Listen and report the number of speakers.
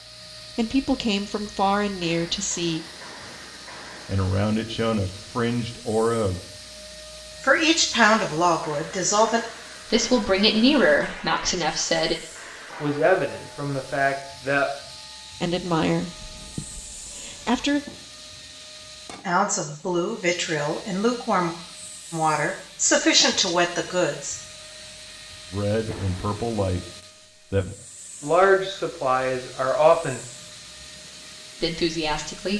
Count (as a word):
five